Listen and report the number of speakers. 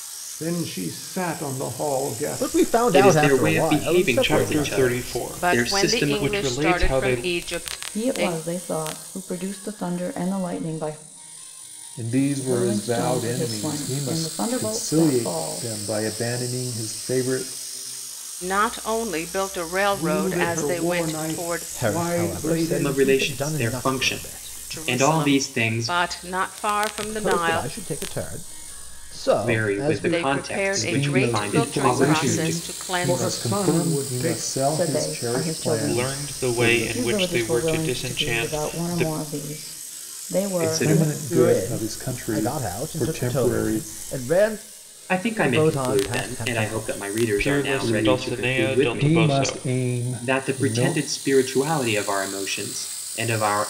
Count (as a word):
seven